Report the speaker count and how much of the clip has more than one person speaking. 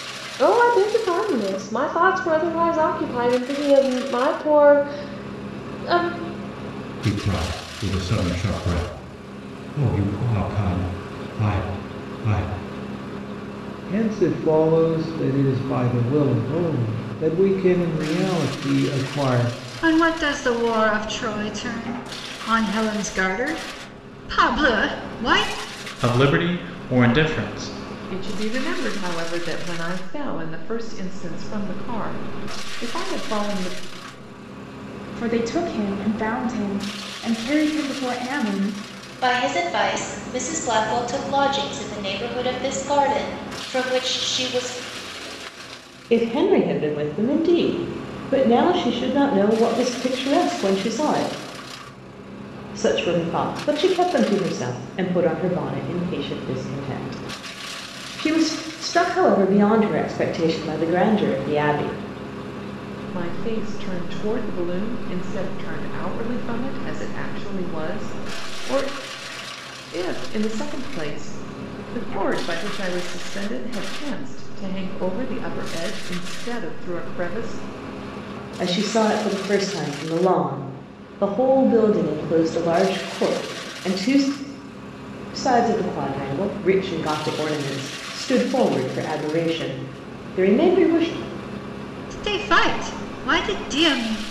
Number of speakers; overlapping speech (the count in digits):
9, no overlap